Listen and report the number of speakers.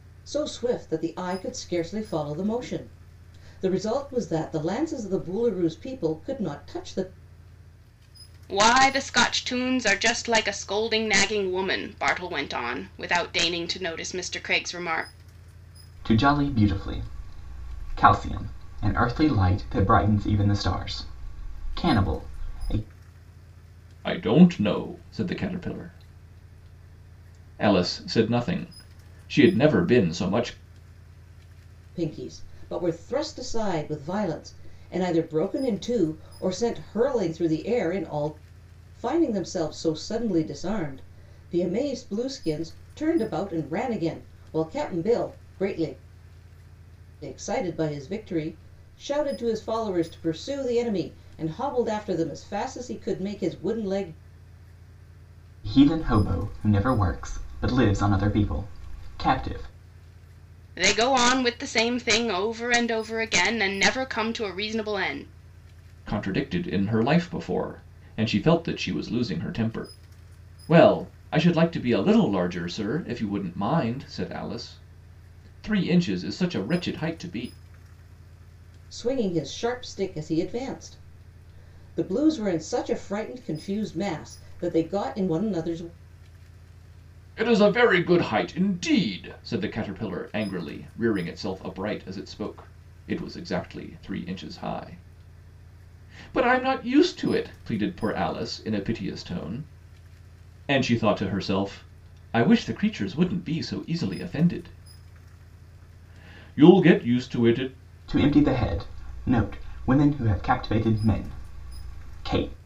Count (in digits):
4